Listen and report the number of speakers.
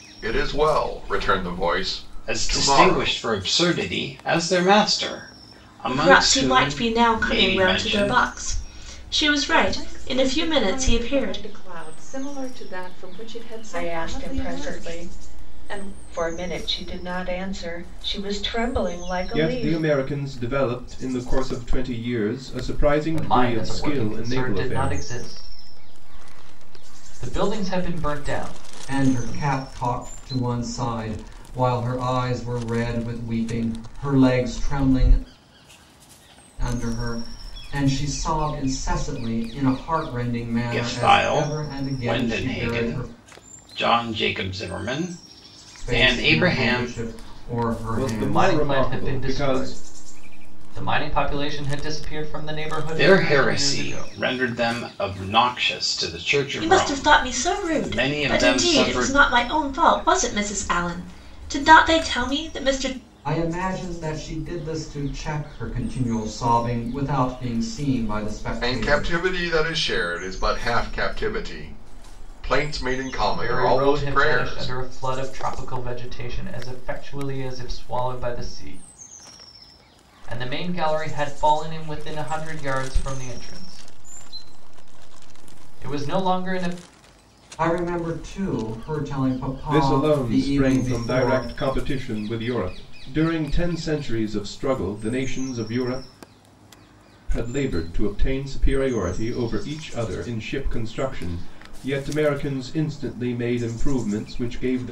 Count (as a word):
eight